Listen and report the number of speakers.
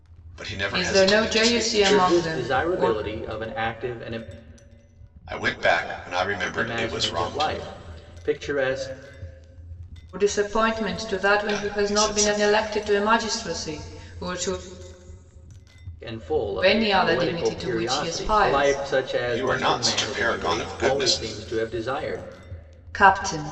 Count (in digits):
3